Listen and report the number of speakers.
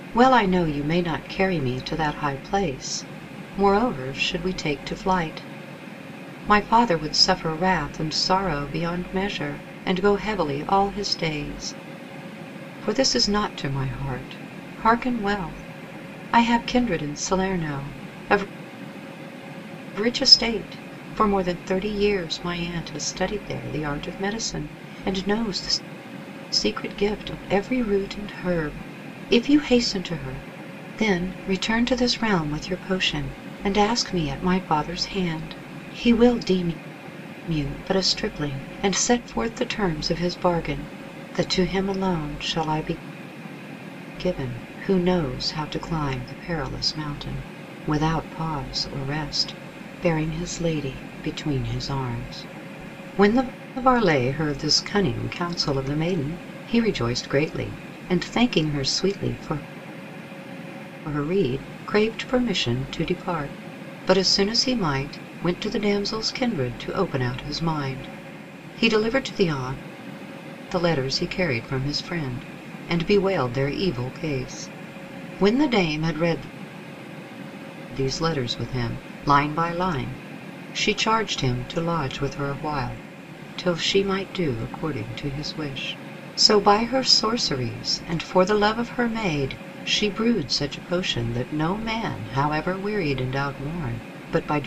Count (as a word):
one